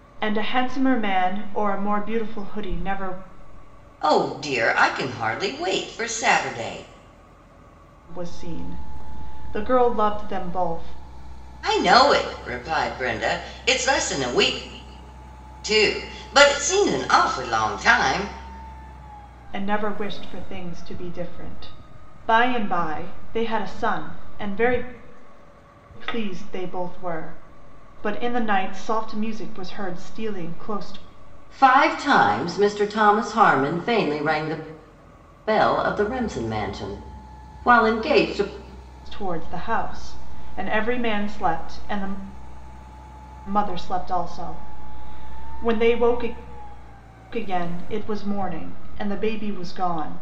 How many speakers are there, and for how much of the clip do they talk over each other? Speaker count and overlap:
two, no overlap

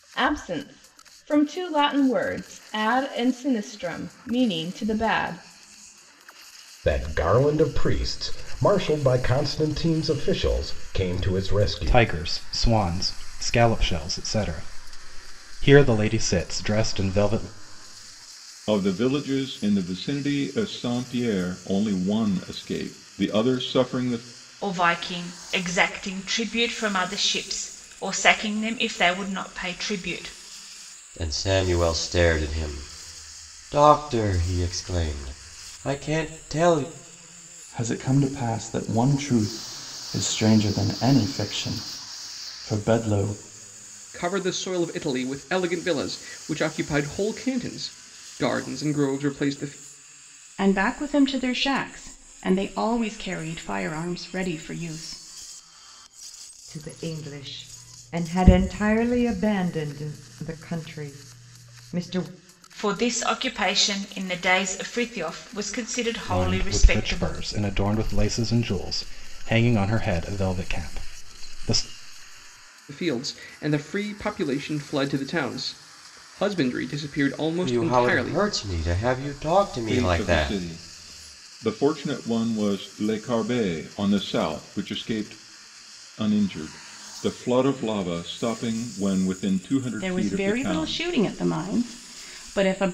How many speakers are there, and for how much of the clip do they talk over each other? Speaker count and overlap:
ten, about 5%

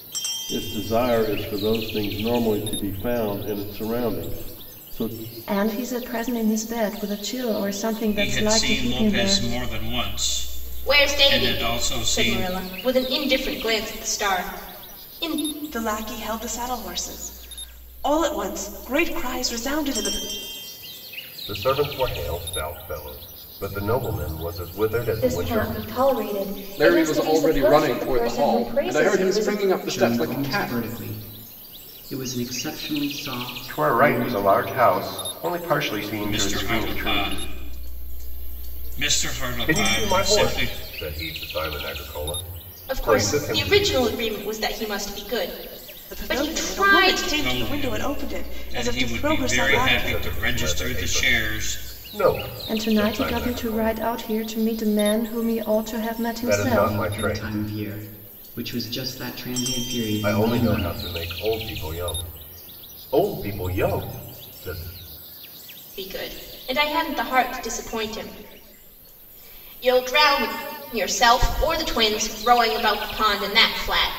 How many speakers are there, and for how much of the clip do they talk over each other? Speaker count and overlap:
ten, about 29%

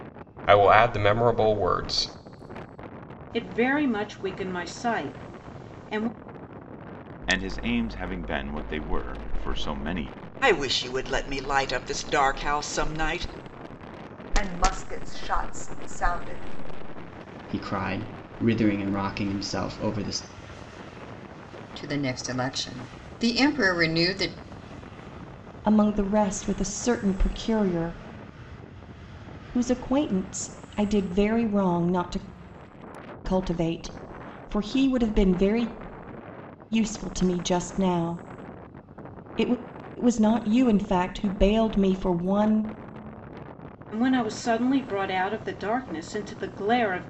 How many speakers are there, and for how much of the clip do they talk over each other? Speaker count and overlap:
eight, no overlap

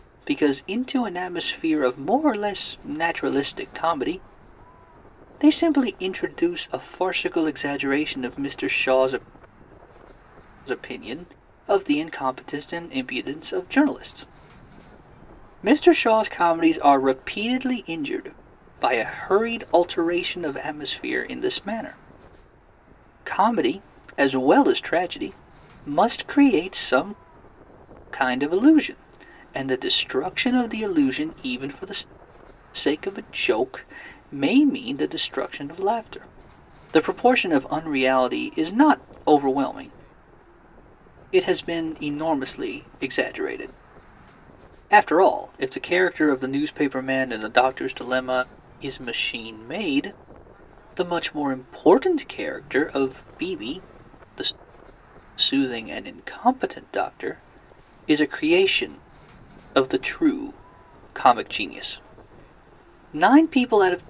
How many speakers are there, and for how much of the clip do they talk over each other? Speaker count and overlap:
one, no overlap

